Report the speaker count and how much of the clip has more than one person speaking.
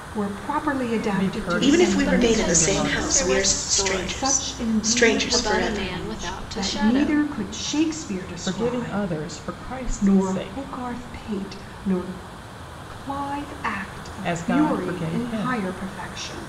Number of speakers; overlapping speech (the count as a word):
four, about 54%